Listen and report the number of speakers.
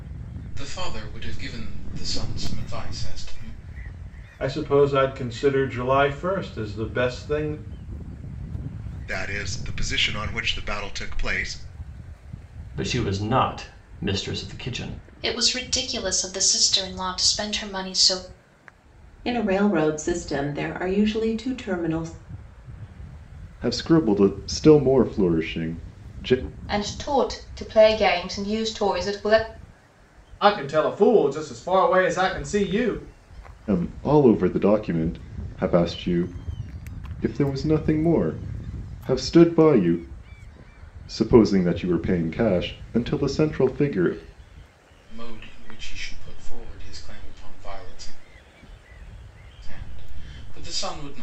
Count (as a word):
nine